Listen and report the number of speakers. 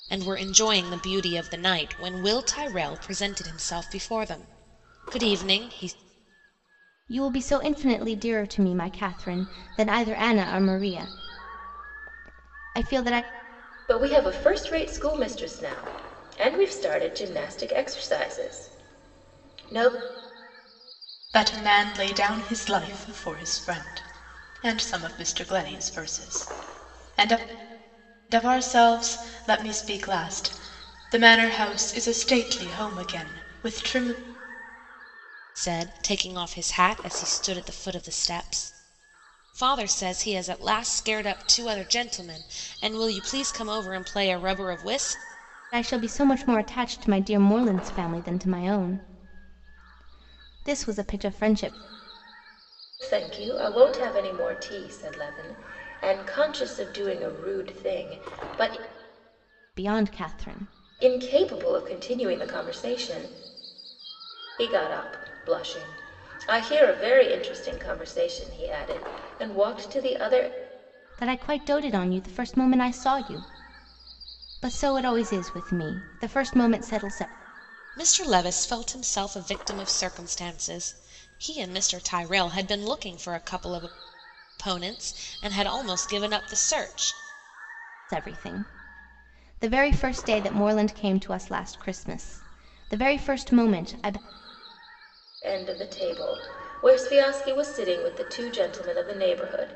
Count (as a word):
four